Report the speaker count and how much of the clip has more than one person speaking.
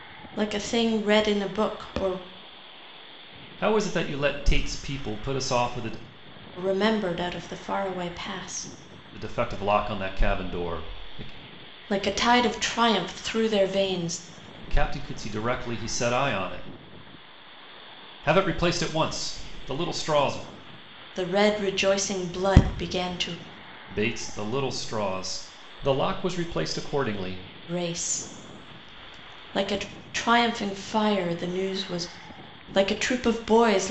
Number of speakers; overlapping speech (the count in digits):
2, no overlap